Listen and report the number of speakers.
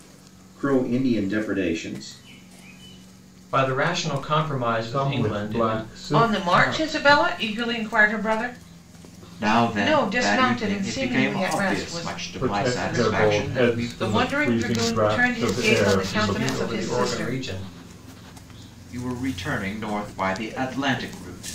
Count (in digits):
5